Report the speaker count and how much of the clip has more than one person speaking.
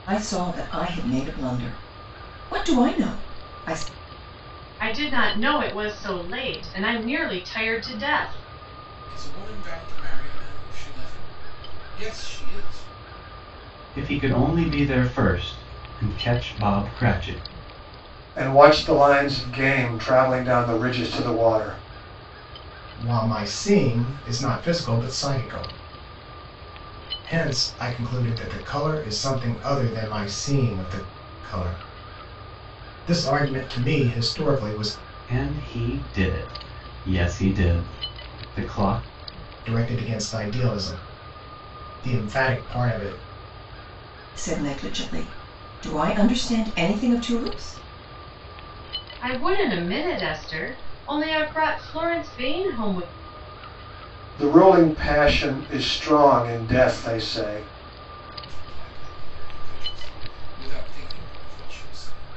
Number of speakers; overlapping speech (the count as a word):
six, no overlap